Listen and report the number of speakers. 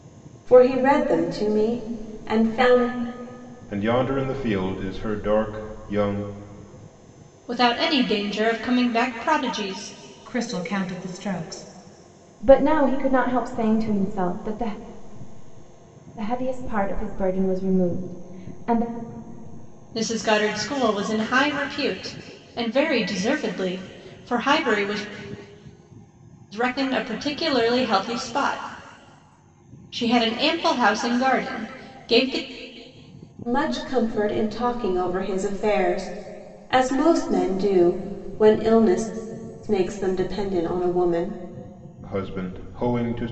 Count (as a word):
five